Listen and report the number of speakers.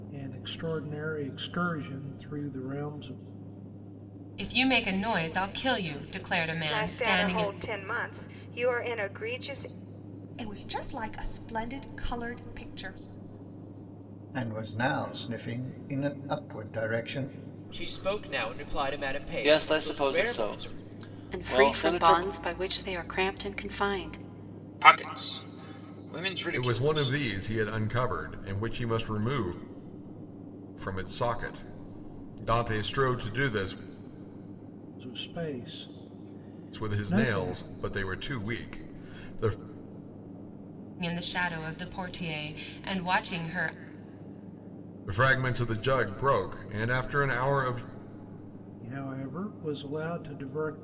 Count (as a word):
ten